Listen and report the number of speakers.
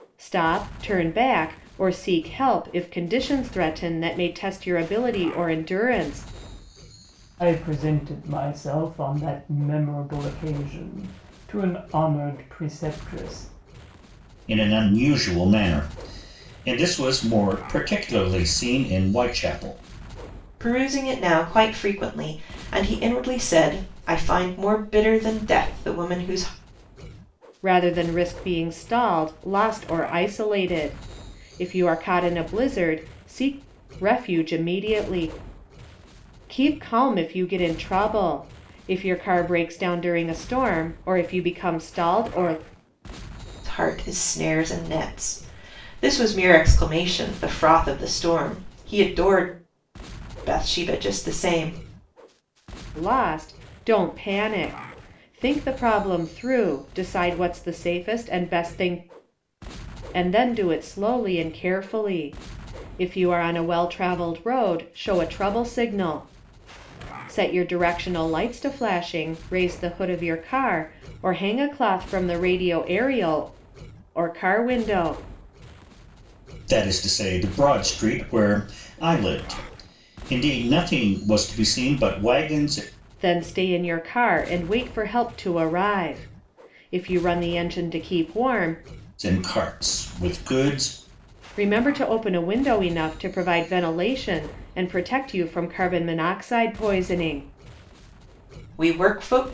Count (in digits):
4